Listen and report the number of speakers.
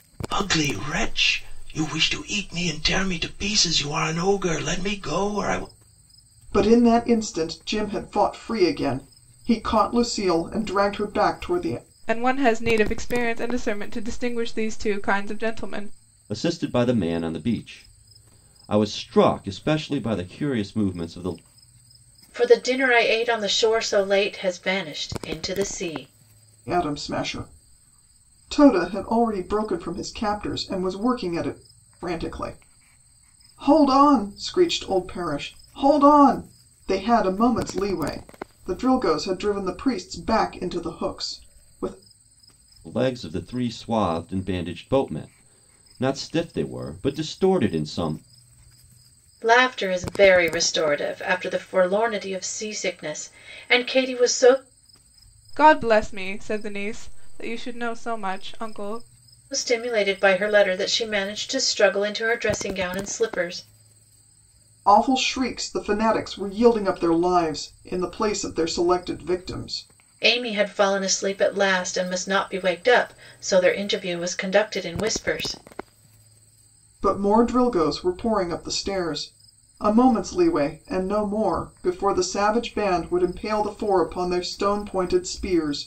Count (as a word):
five